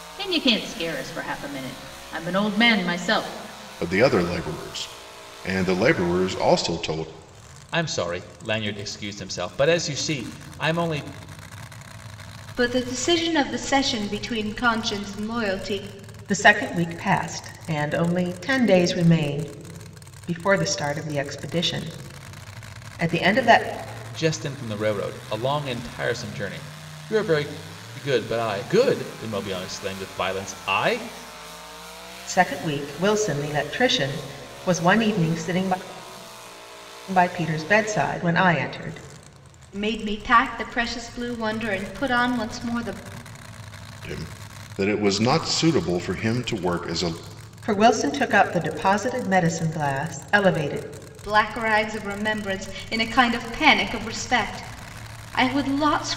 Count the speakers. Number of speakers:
5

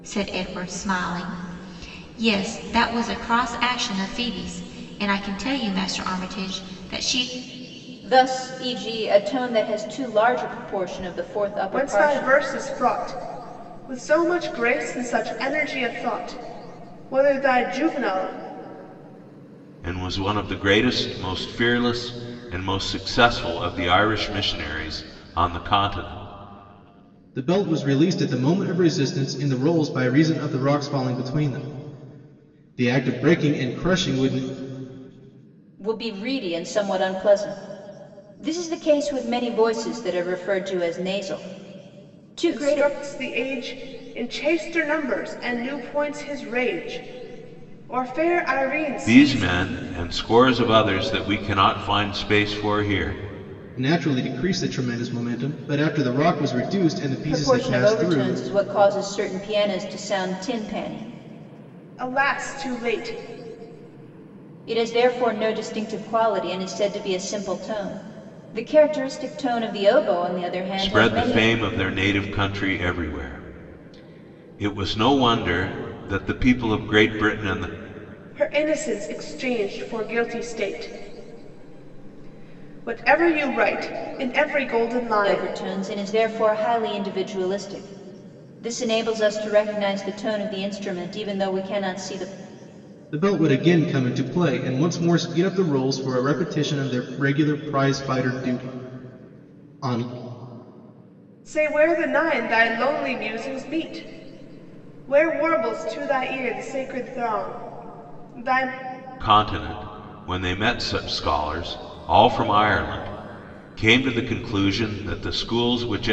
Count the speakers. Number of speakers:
5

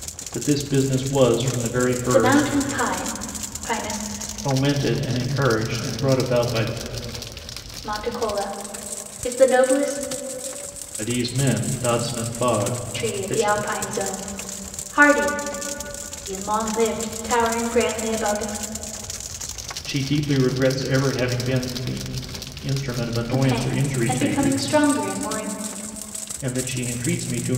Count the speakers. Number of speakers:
2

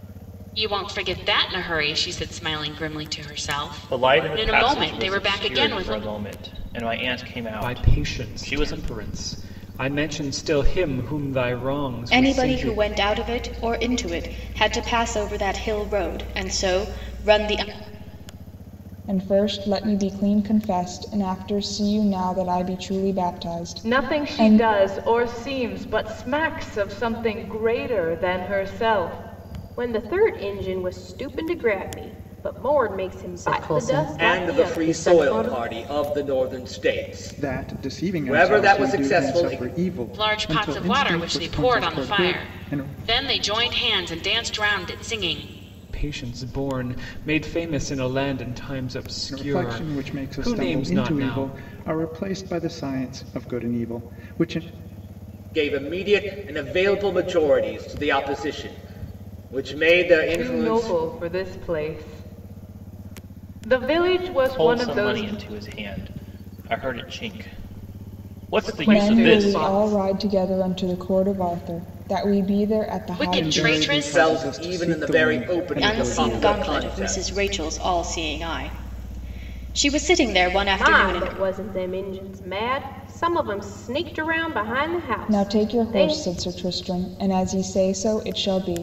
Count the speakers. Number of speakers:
10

